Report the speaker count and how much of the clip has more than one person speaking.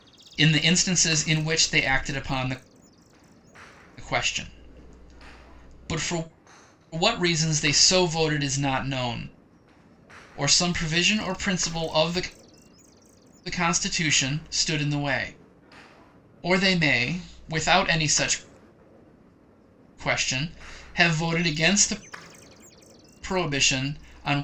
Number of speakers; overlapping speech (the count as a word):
one, no overlap